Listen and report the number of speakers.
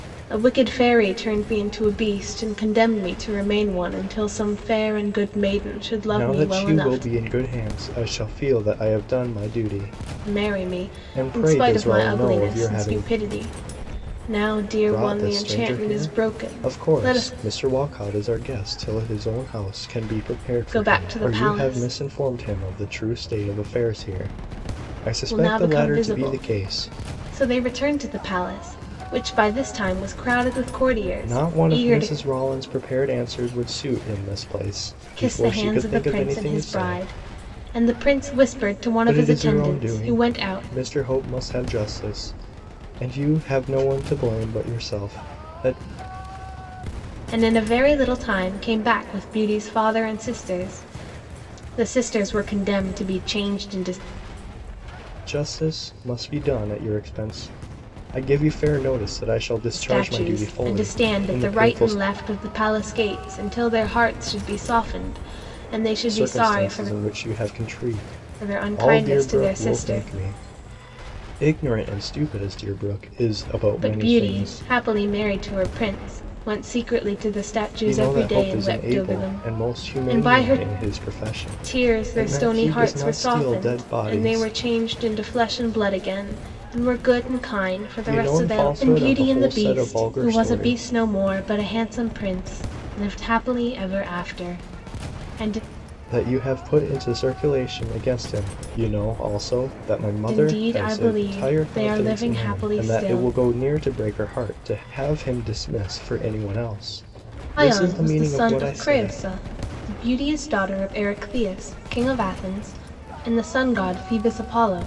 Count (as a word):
two